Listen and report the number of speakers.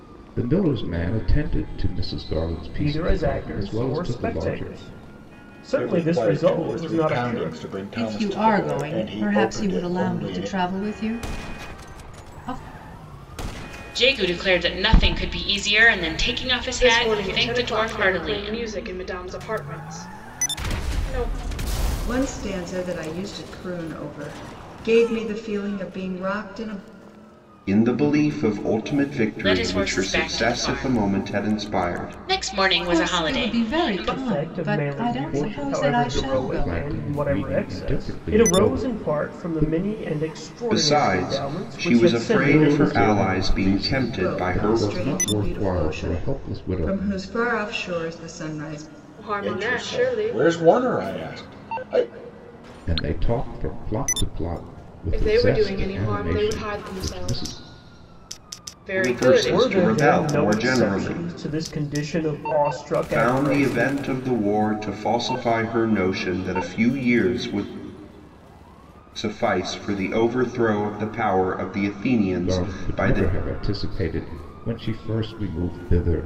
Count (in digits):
8